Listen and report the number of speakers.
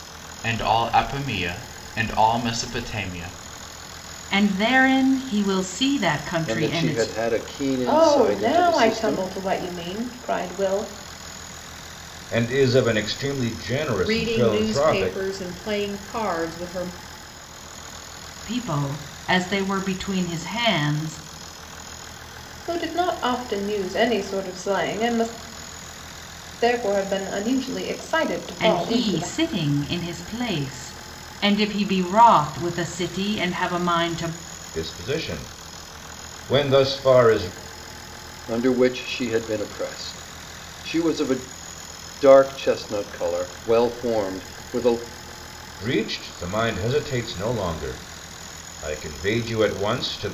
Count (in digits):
6